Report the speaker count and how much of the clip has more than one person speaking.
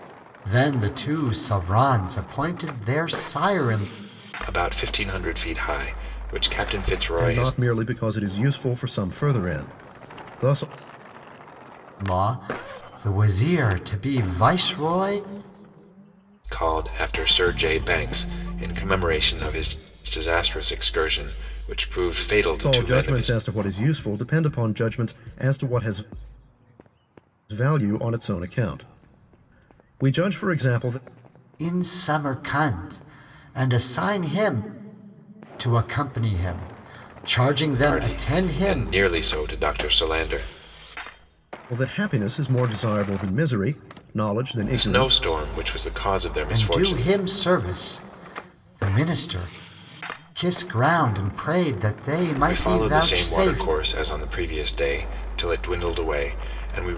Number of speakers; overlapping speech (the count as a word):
three, about 9%